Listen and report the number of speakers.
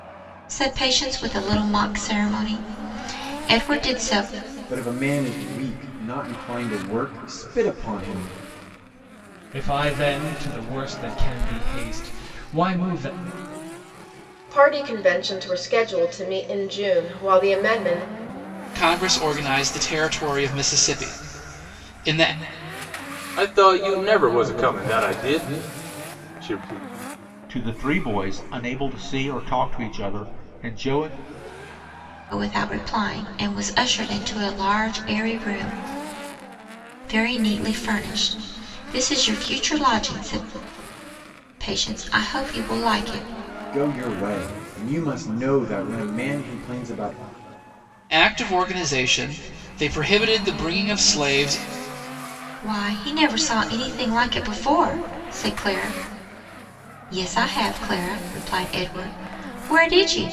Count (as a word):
seven